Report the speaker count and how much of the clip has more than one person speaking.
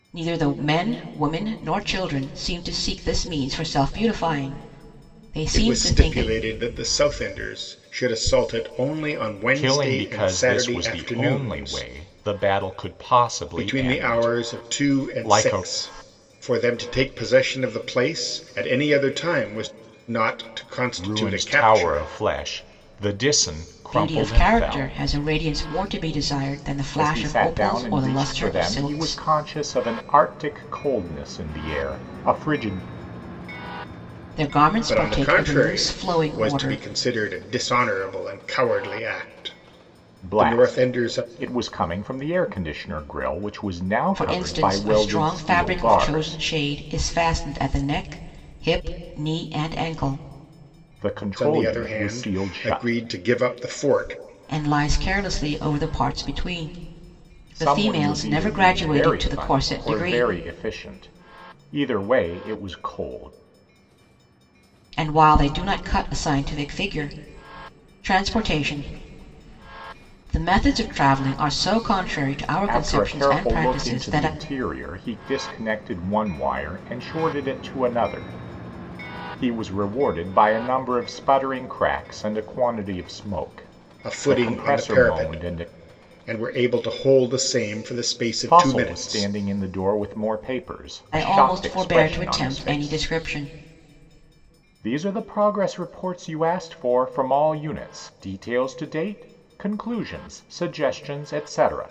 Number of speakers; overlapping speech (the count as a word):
three, about 25%